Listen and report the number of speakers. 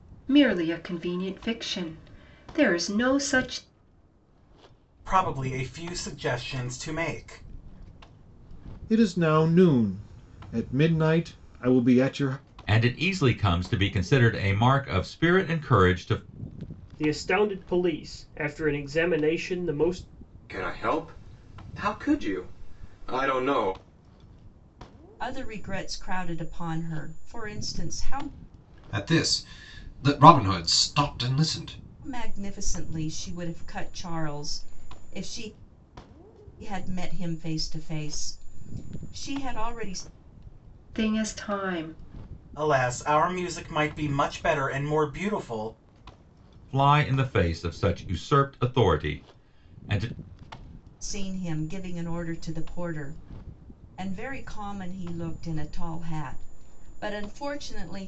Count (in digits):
8